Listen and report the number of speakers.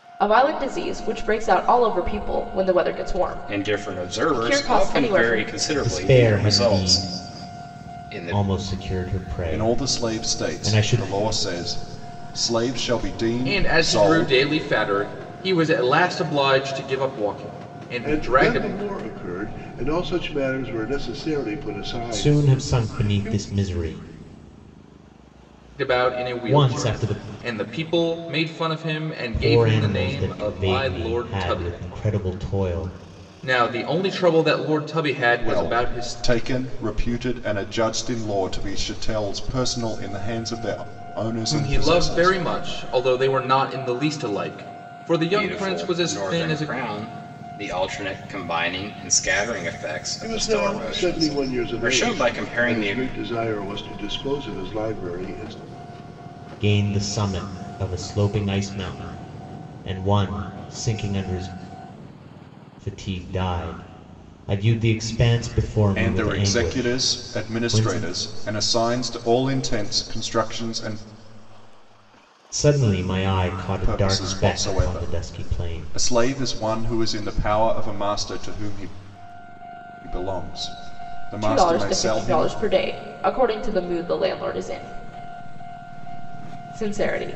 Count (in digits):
6